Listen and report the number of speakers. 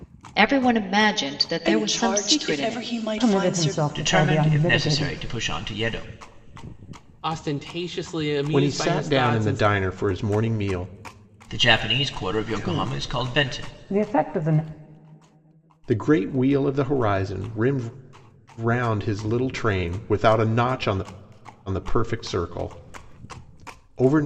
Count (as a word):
six